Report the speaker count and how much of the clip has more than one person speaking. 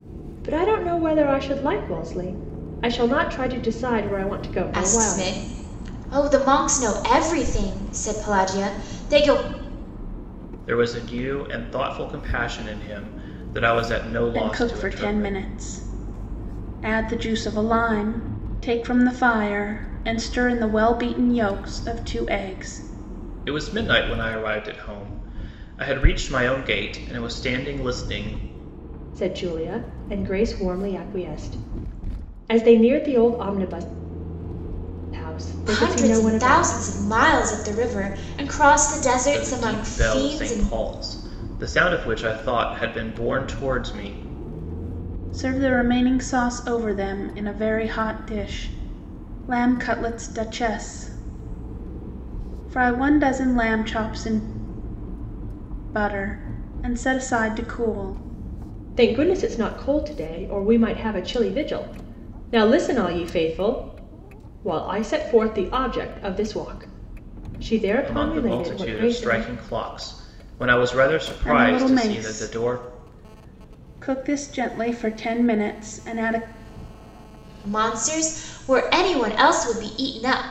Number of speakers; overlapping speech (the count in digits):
4, about 9%